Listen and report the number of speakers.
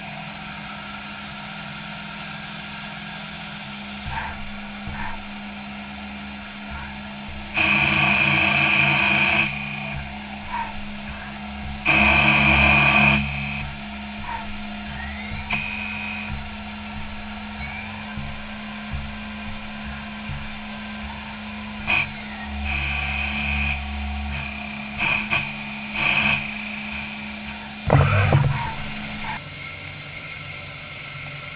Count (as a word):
zero